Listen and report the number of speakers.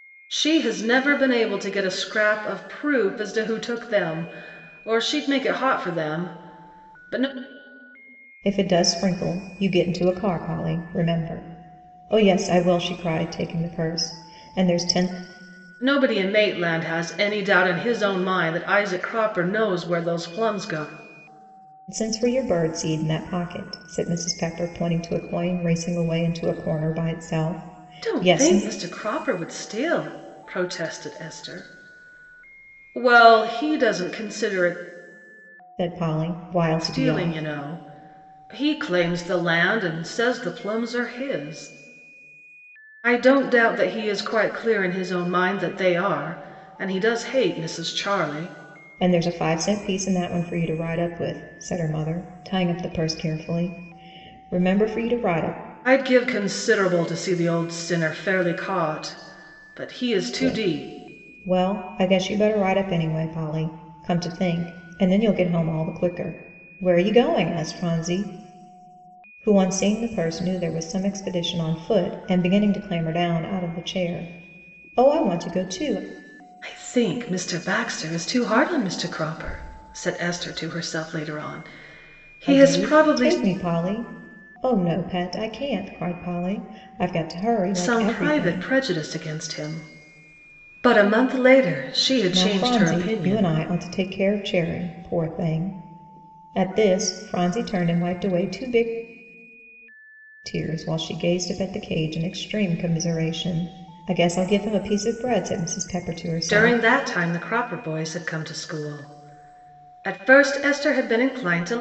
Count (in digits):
2